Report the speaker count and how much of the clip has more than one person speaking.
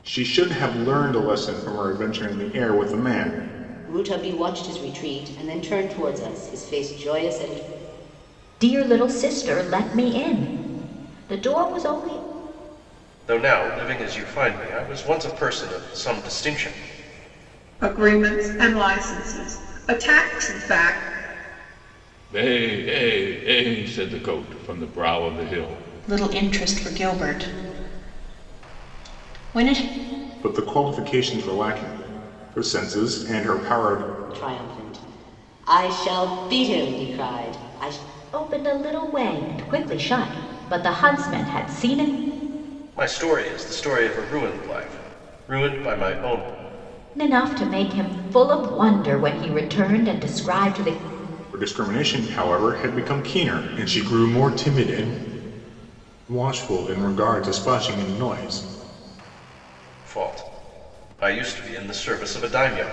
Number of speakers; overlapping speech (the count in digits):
7, no overlap